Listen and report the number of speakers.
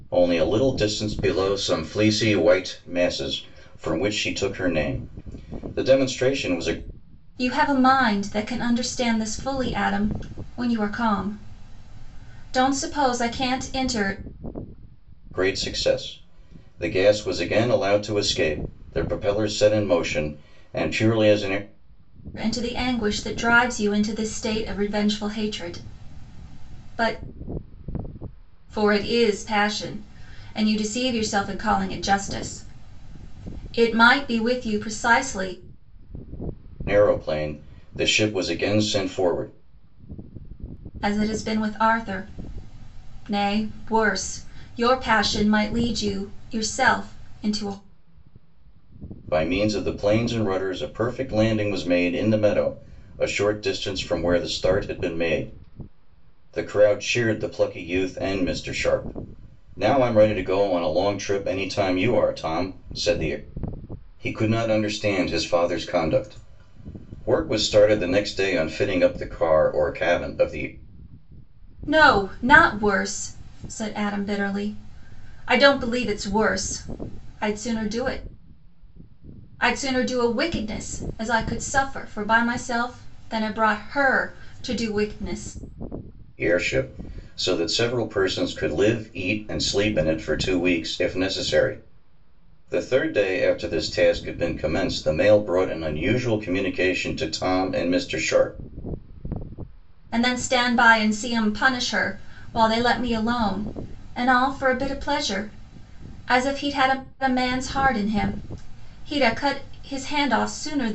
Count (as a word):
two